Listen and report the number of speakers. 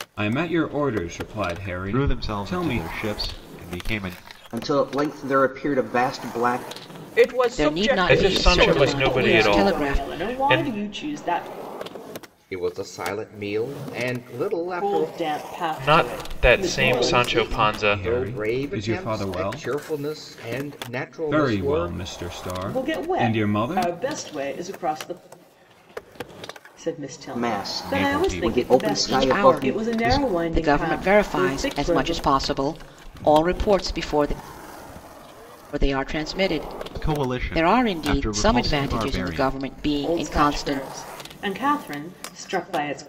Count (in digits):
8